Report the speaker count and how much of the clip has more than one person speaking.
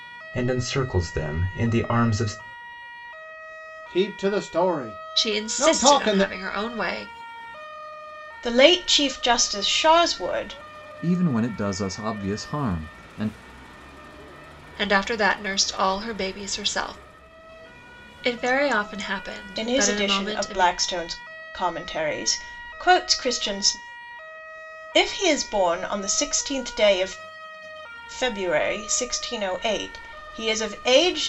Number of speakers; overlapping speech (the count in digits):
5, about 7%